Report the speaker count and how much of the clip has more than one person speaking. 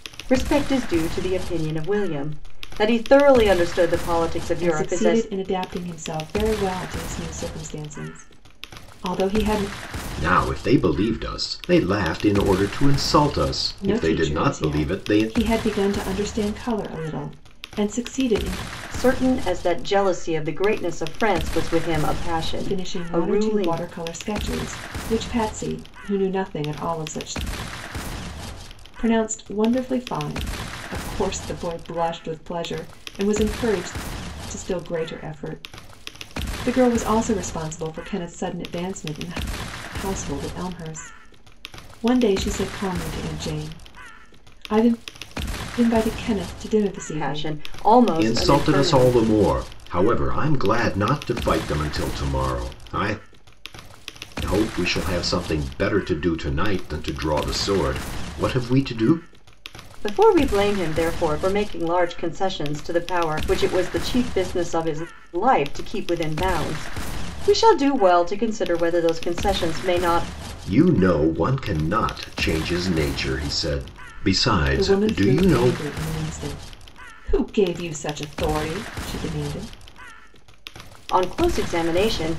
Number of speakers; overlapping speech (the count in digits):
3, about 7%